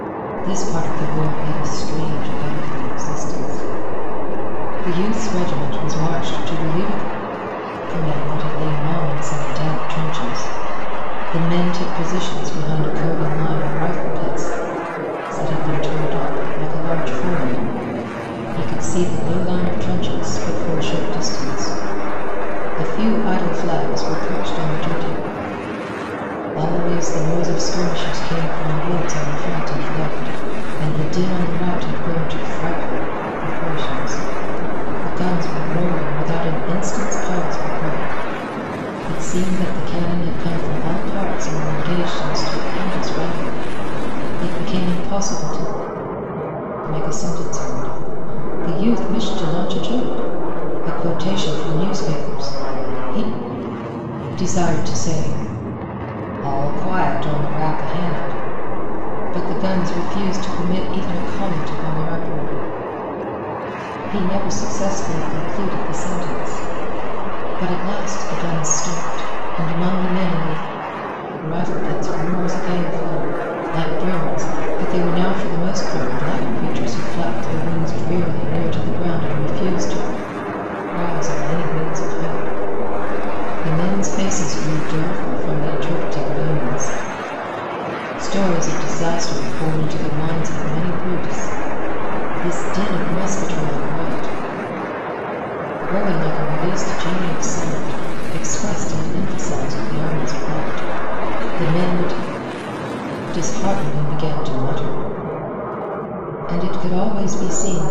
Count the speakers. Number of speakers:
1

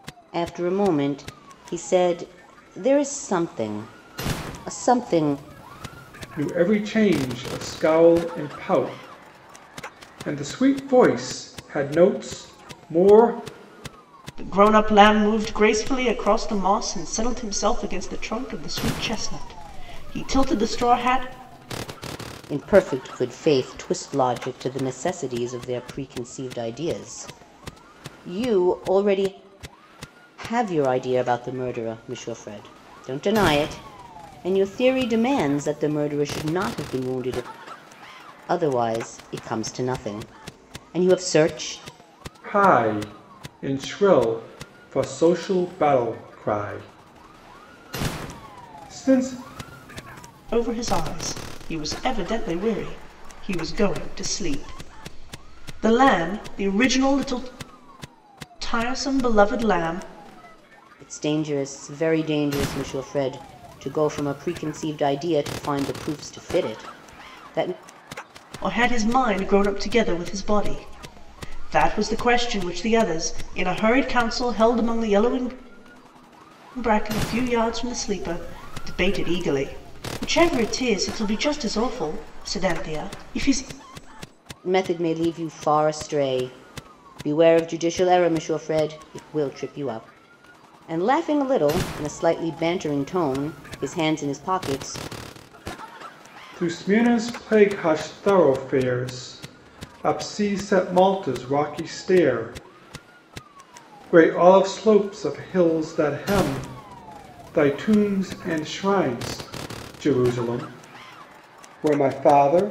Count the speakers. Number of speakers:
3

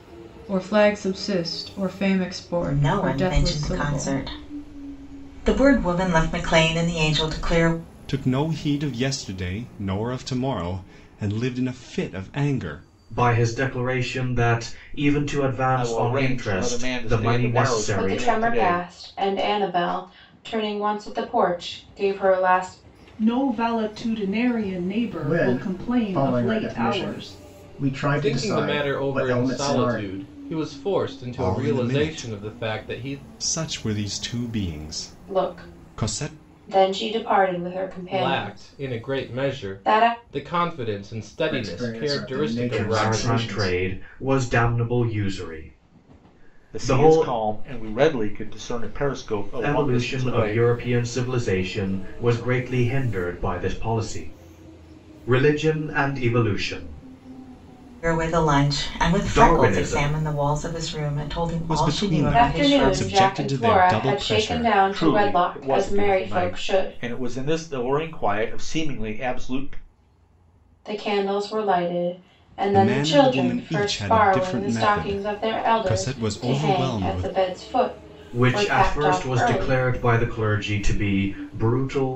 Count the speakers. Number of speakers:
9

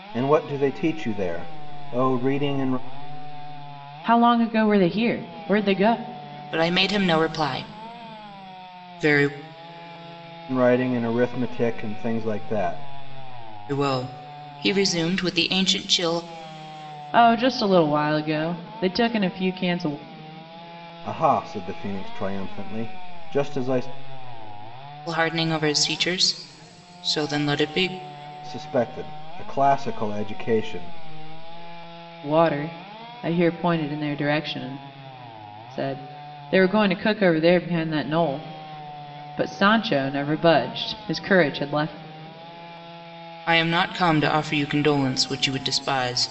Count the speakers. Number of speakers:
3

